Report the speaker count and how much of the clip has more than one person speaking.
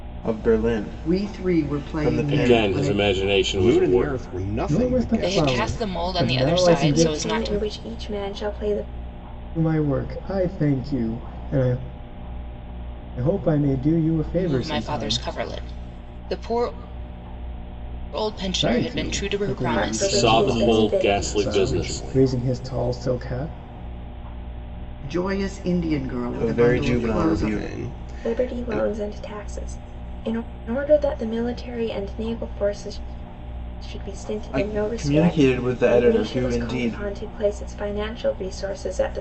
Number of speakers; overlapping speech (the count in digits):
7, about 38%